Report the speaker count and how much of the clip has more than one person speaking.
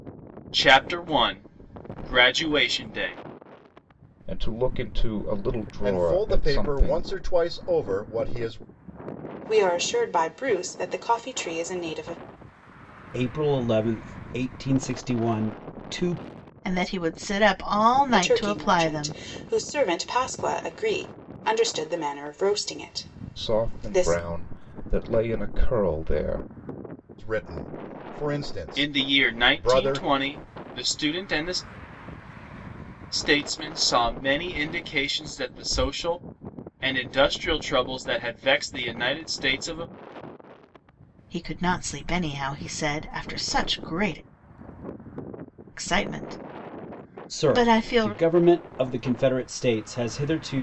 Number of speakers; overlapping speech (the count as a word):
six, about 11%